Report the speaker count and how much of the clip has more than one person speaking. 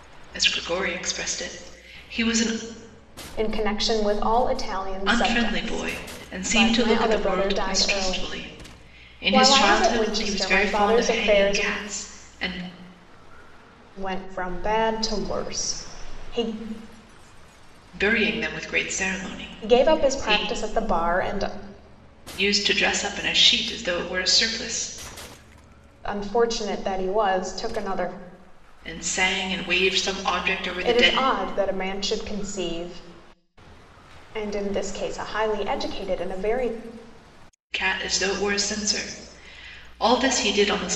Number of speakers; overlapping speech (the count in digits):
2, about 15%